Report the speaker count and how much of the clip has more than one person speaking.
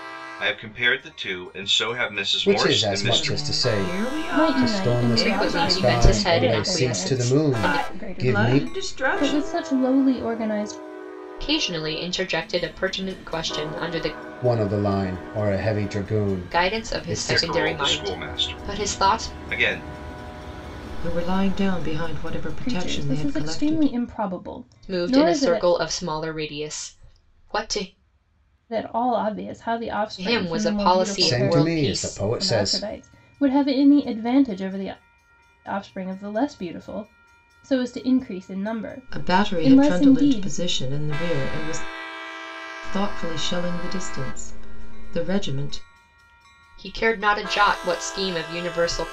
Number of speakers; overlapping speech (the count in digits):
5, about 33%